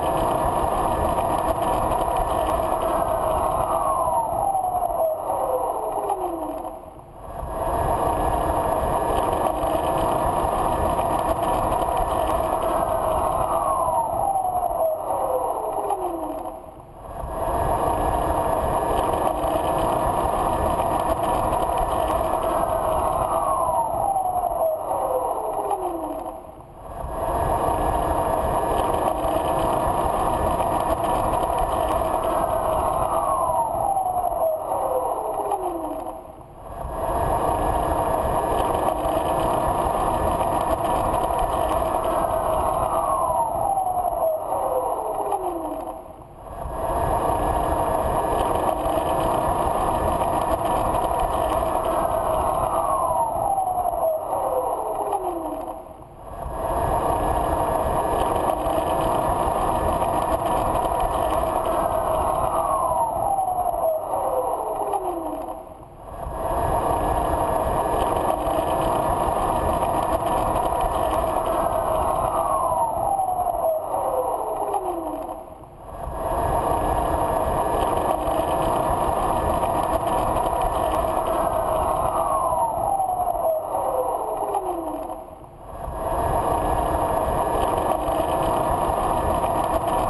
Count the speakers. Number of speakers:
0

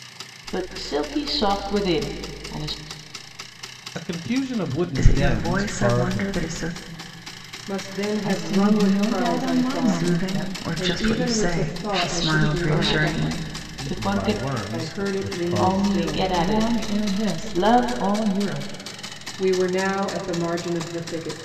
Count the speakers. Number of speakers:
5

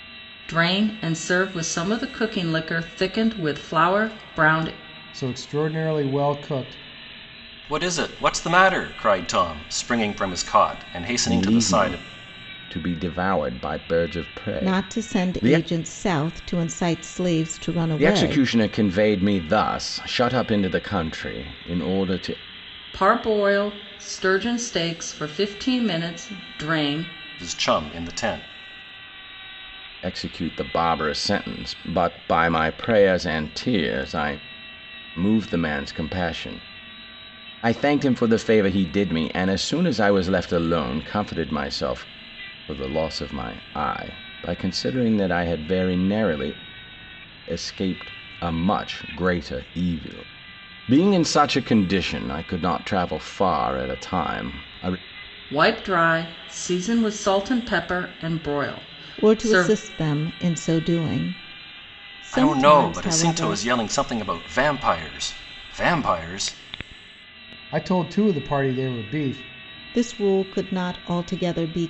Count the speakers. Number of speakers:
5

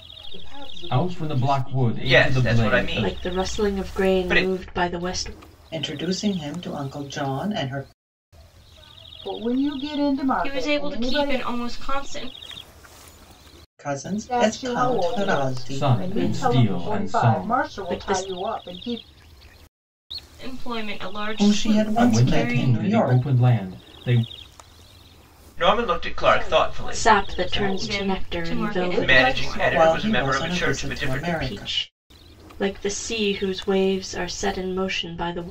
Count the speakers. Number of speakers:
7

